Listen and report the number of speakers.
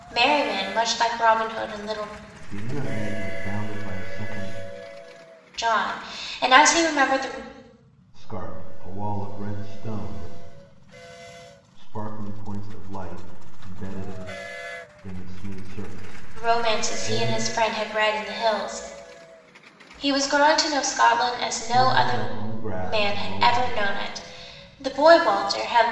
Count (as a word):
two